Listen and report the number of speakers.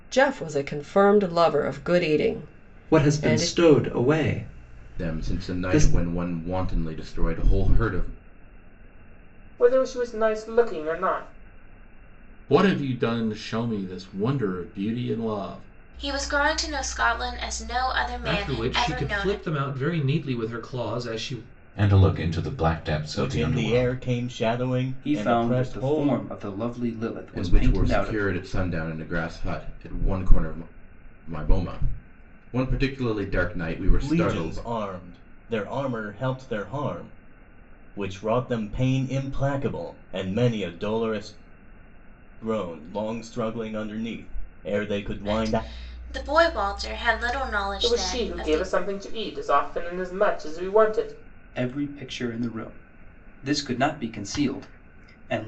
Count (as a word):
ten